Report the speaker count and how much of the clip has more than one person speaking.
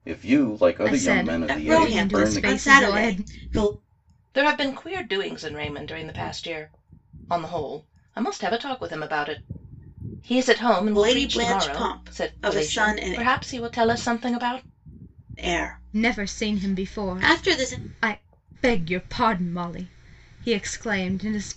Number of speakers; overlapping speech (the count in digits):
4, about 30%